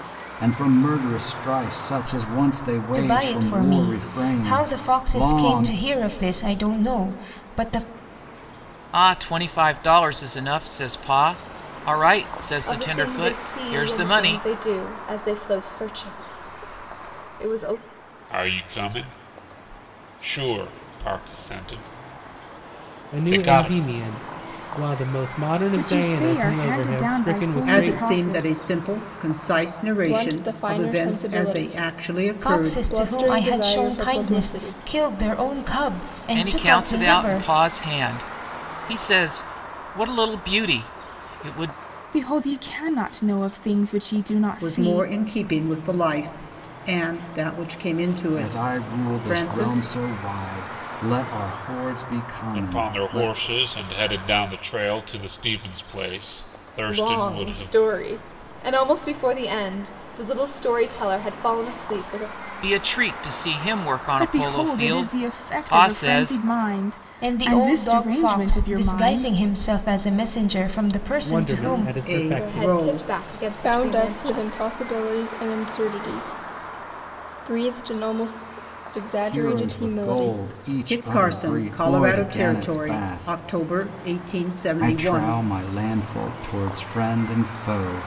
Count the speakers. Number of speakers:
9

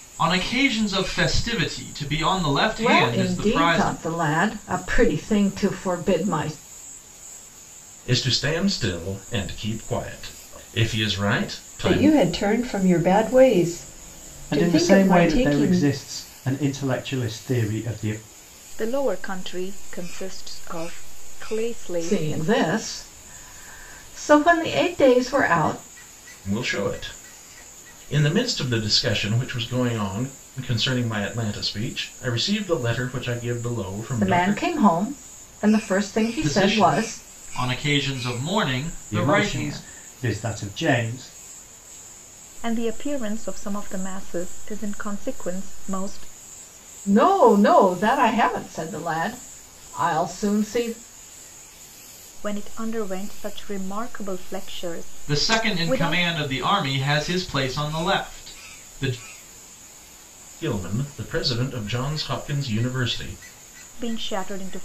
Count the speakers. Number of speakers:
6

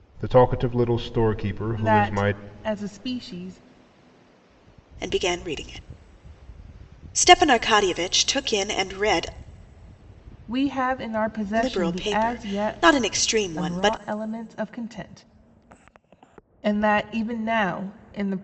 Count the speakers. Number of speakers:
3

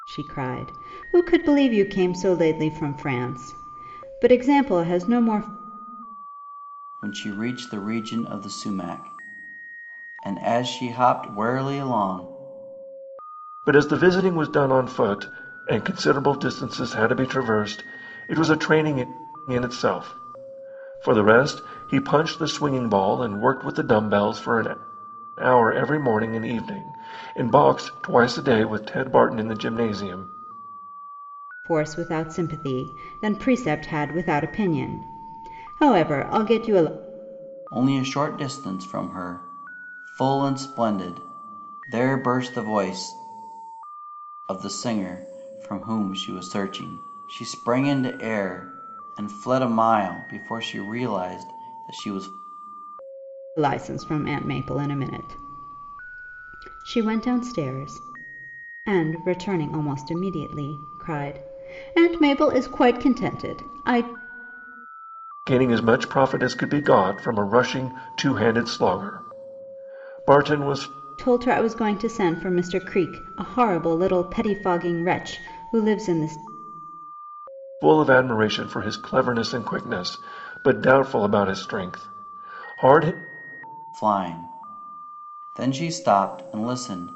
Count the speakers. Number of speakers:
3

